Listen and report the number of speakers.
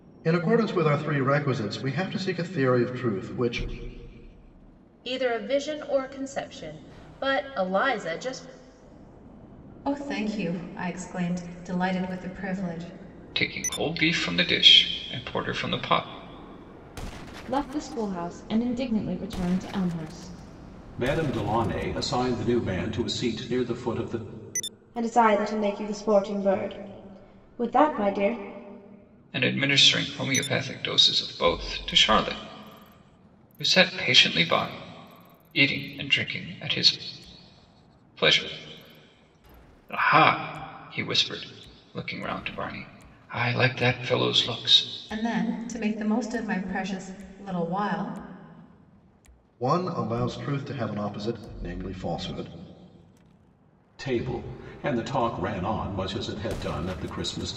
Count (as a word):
seven